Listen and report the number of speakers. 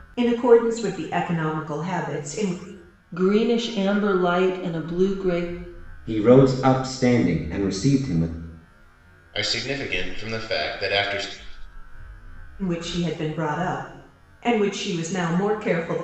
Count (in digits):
4